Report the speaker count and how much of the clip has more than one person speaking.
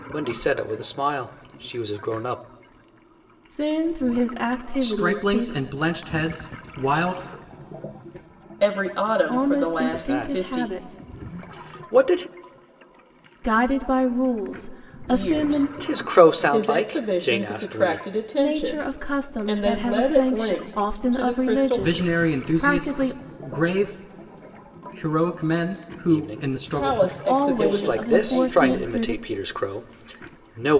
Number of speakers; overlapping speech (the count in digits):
4, about 44%